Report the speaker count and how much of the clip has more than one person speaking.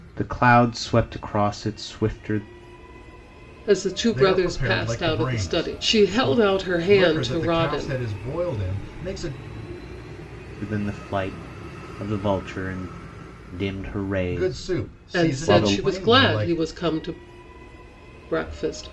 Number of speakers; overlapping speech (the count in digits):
3, about 30%